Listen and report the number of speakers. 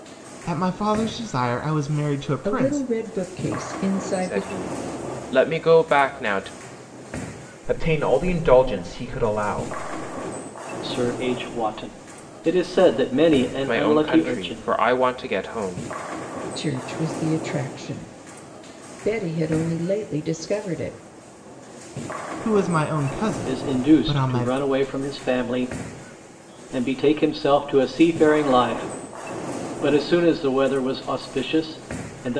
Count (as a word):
five